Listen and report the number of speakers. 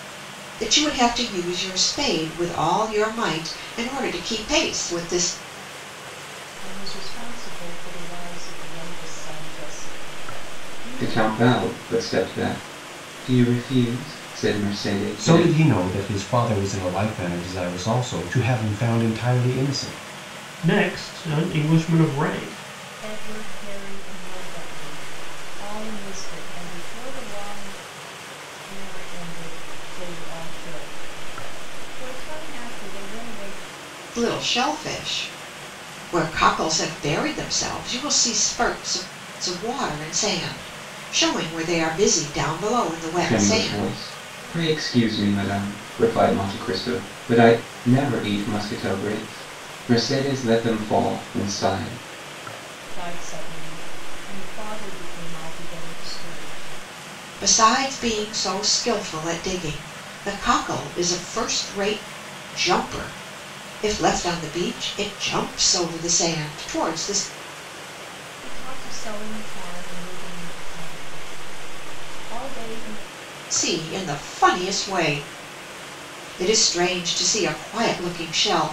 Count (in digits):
5